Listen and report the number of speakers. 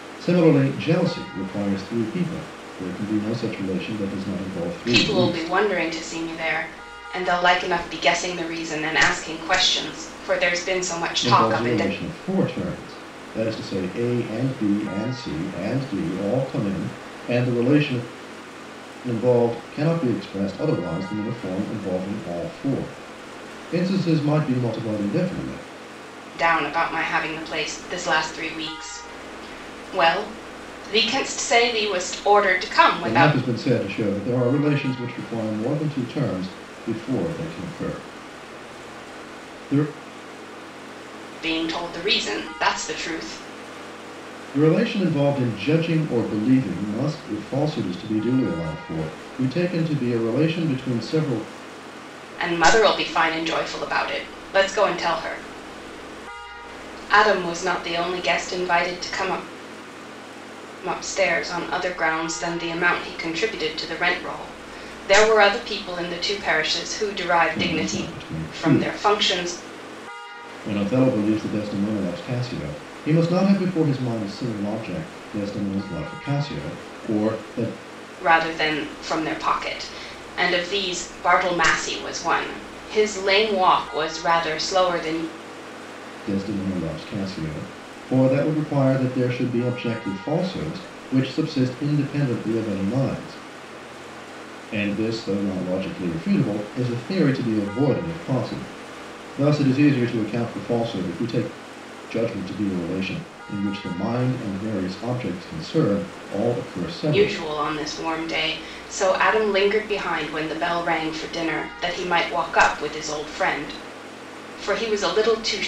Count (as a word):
two